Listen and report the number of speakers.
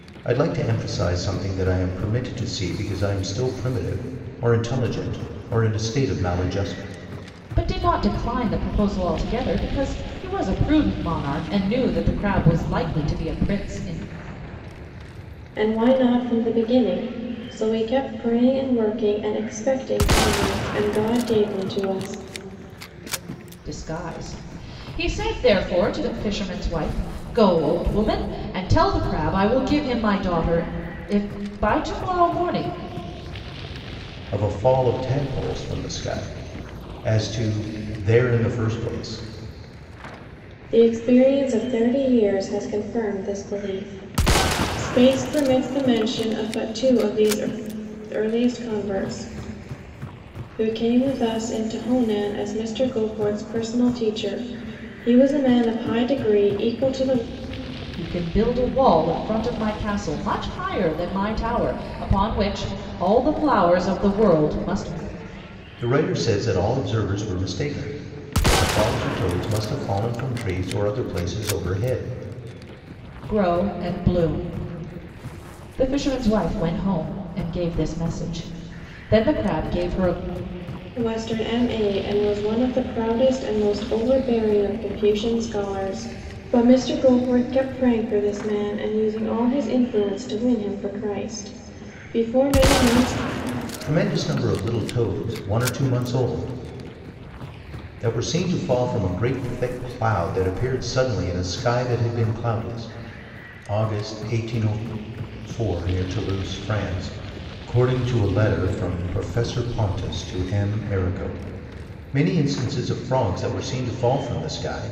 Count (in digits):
3